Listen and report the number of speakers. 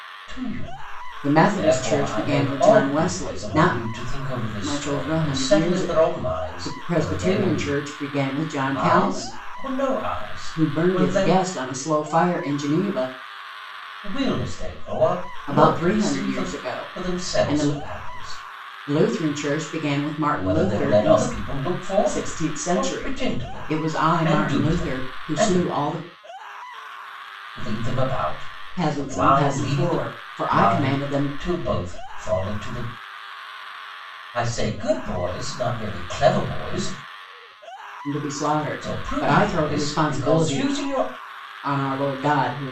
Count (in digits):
2